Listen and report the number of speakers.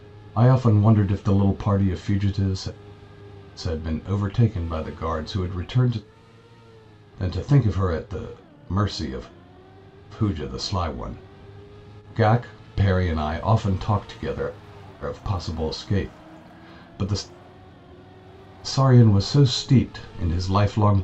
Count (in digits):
1